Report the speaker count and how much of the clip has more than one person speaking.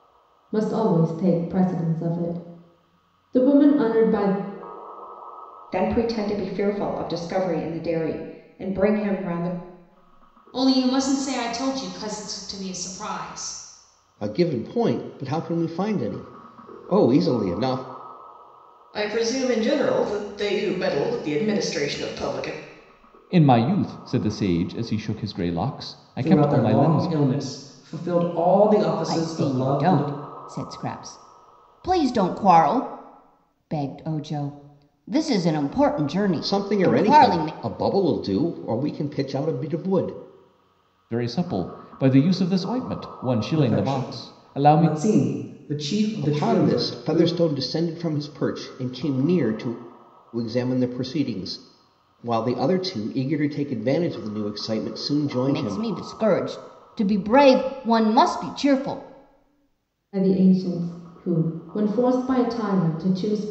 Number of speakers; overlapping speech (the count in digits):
8, about 9%